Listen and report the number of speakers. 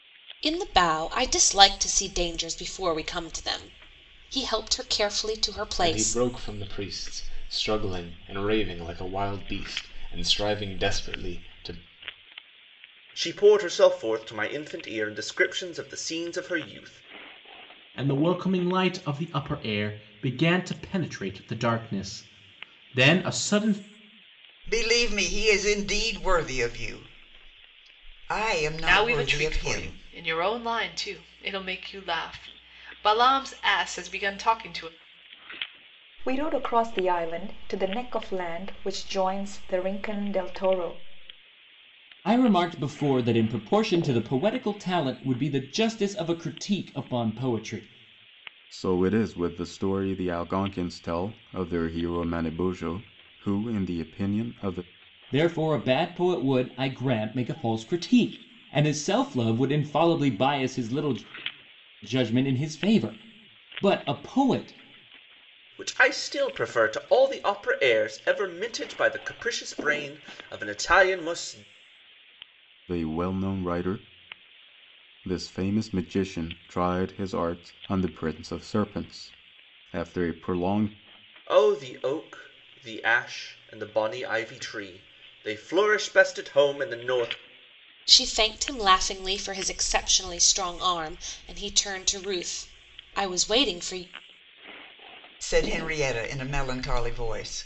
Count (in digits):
9